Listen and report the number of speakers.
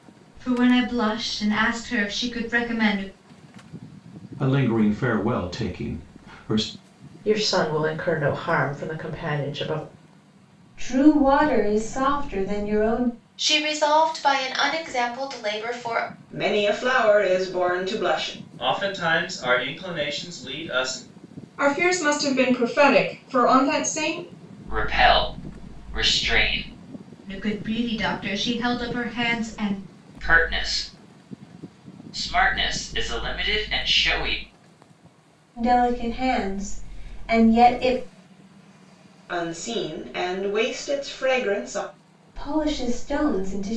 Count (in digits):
9